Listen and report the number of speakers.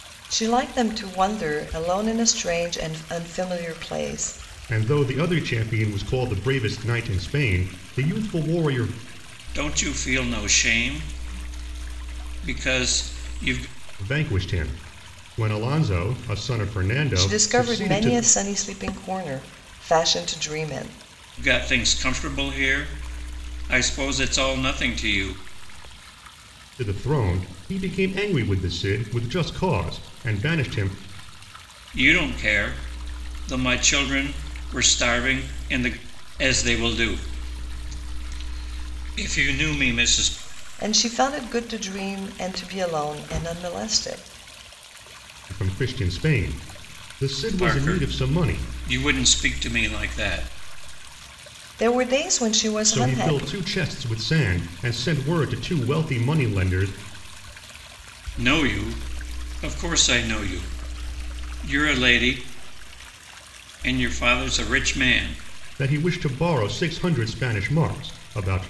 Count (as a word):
three